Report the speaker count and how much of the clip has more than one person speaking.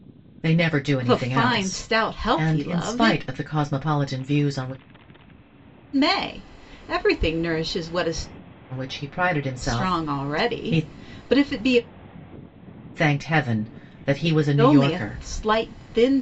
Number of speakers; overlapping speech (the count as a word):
two, about 23%